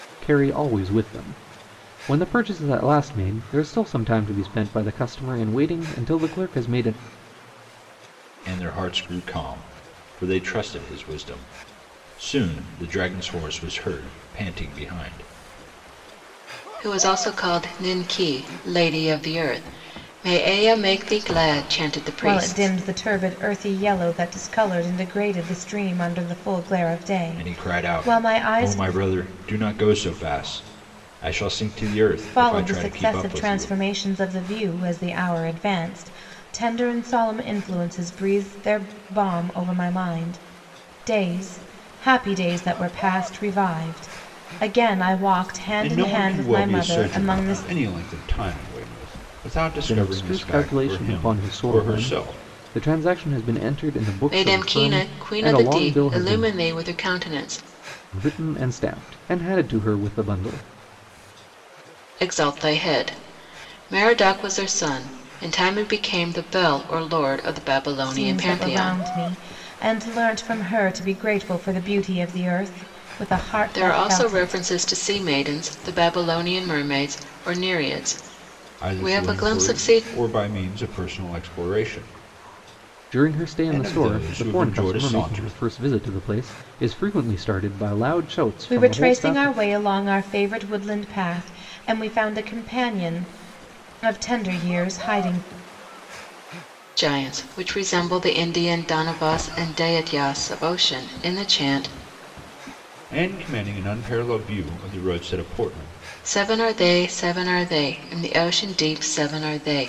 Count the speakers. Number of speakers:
four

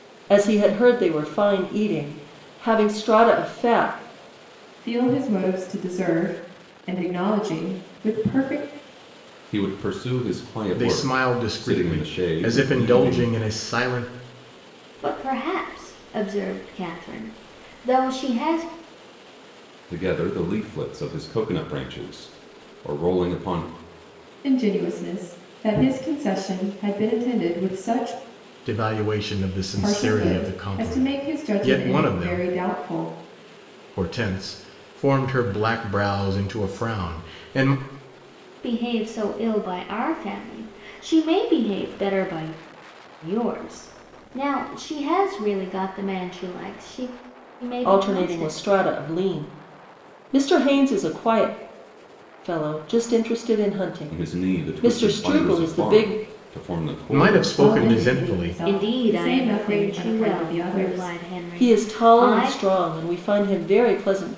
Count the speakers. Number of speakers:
five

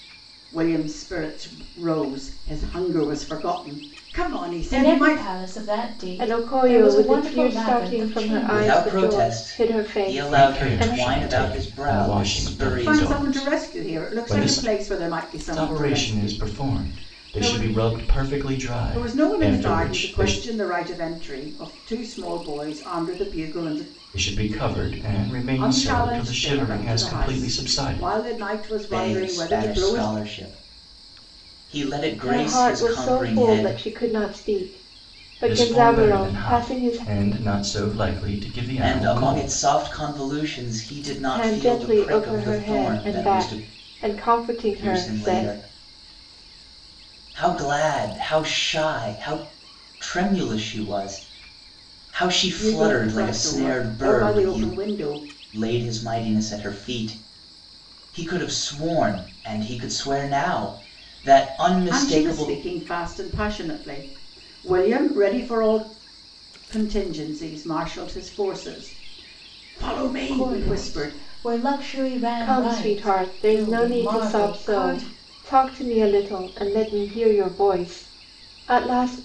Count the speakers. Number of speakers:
five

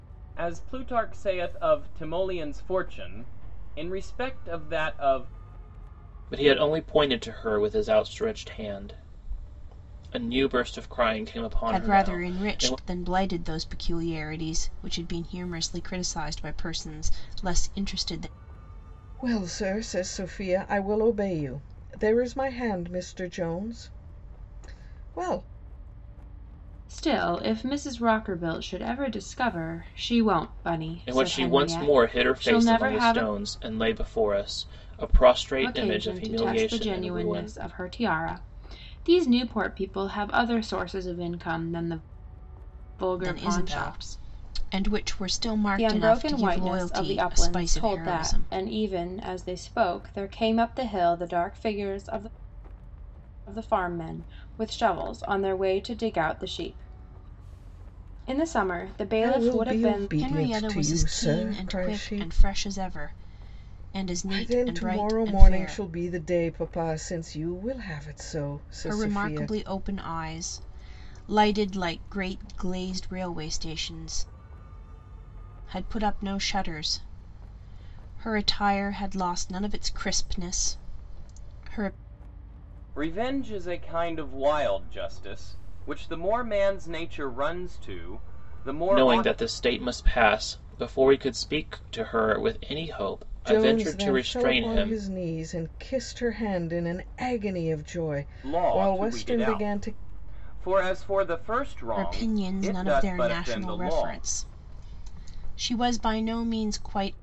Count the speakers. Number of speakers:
five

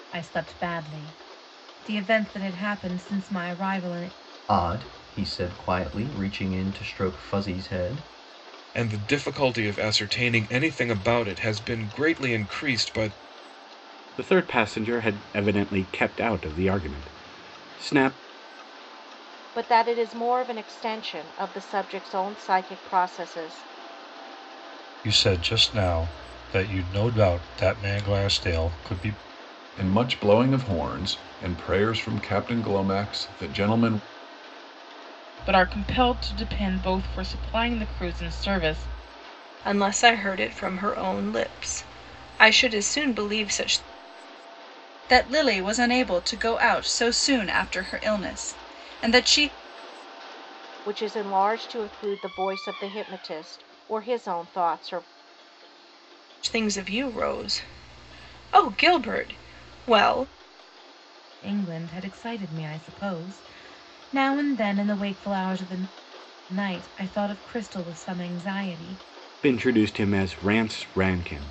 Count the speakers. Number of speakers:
ten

